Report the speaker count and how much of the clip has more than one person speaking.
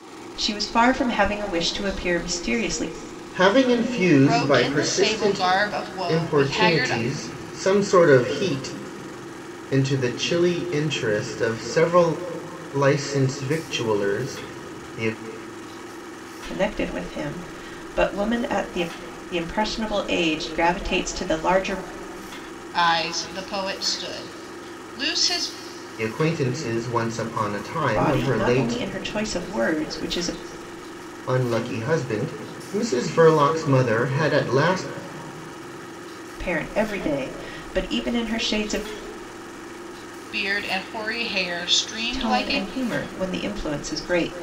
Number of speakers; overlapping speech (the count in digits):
3, about 8%